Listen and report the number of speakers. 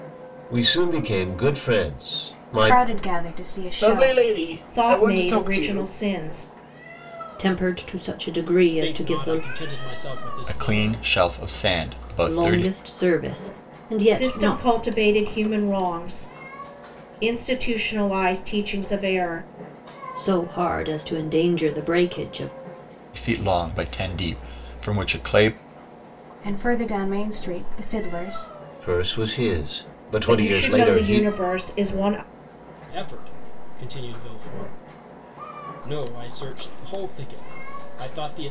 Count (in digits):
7